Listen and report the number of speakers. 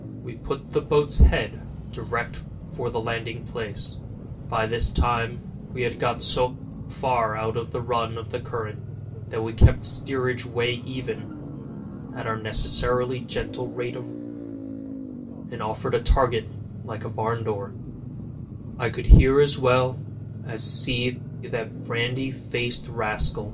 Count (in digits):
1